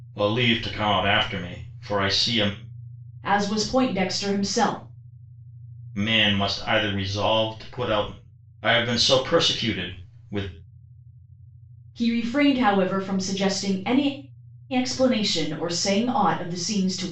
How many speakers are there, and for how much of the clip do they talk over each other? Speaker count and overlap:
two, no overlap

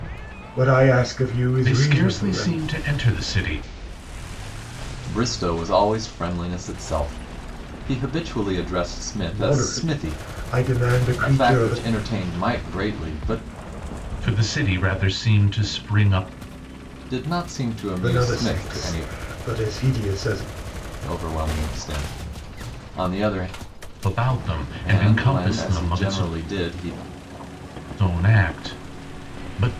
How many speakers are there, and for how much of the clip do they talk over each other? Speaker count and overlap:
three, about 17%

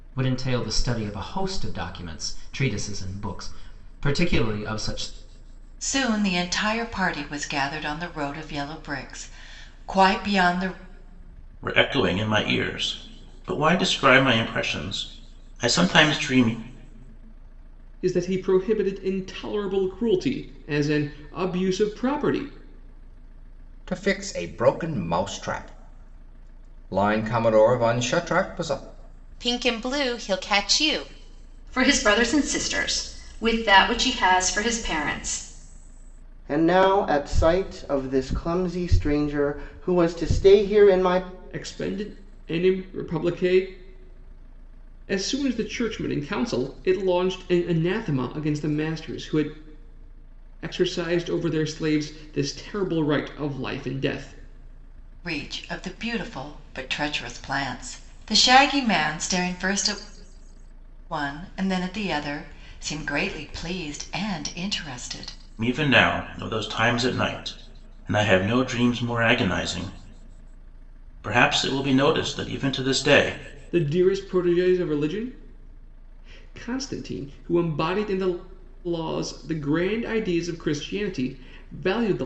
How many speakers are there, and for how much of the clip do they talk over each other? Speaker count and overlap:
eight, no overlap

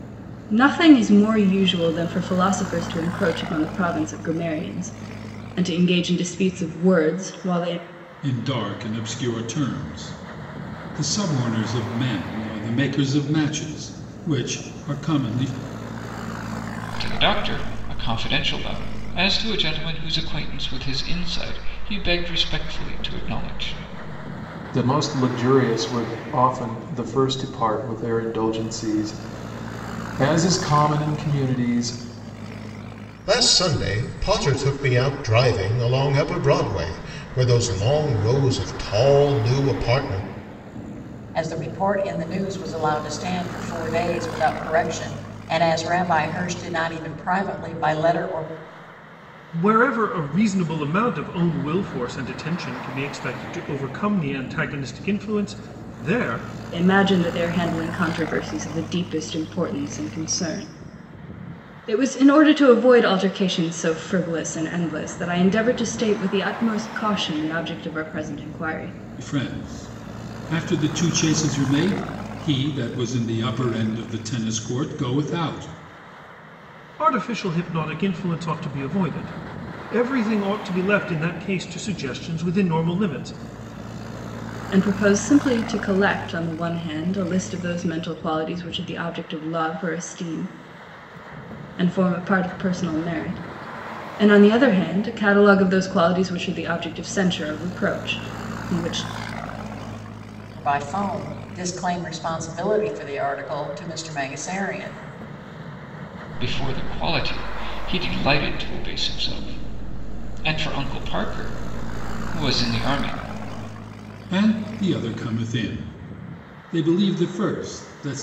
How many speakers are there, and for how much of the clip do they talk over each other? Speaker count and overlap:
seven, no overlap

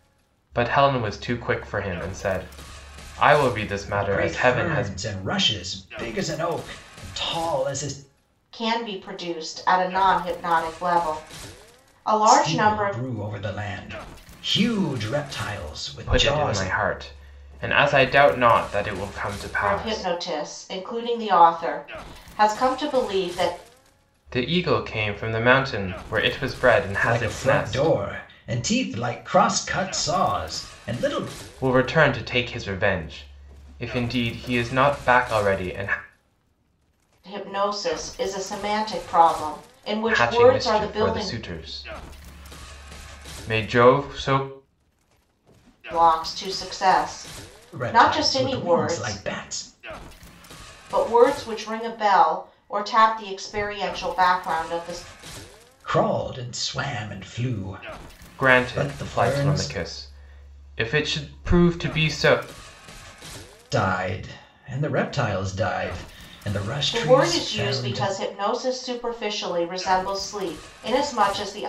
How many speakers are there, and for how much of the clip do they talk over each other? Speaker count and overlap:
three, about 13%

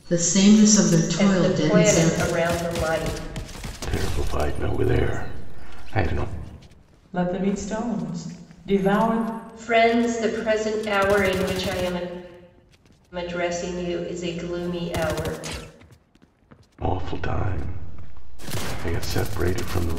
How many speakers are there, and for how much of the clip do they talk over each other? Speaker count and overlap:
four, about 5%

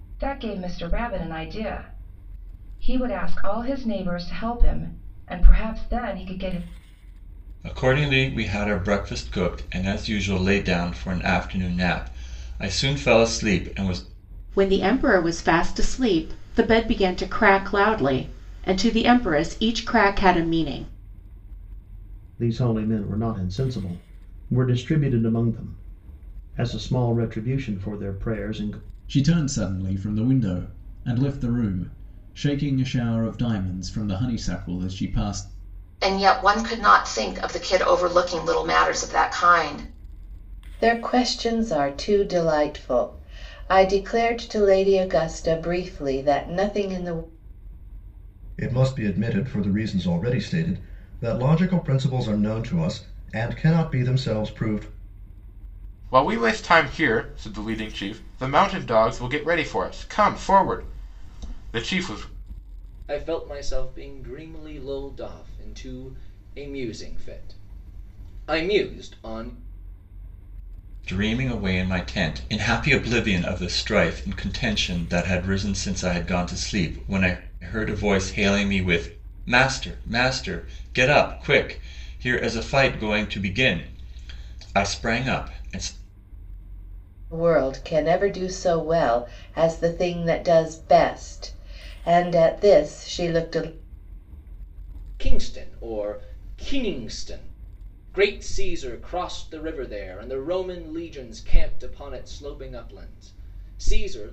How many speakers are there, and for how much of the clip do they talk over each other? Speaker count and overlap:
ten, no overlap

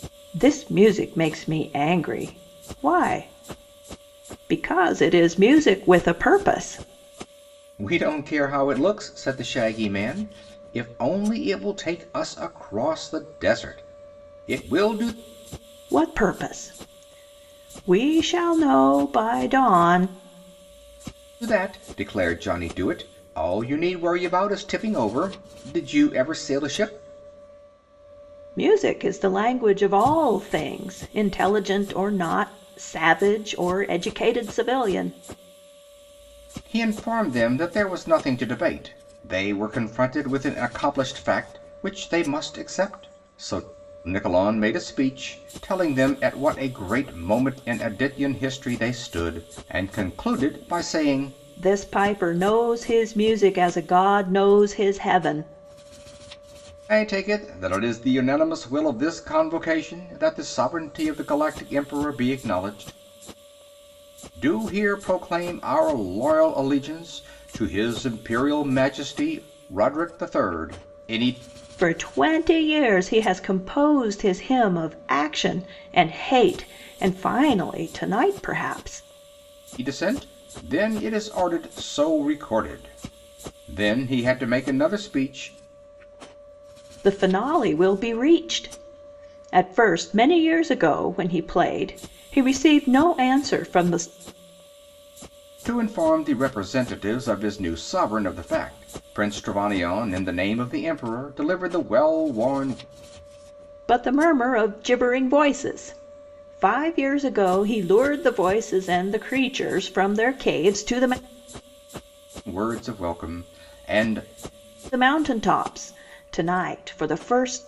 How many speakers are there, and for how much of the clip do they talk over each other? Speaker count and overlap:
two, no overlap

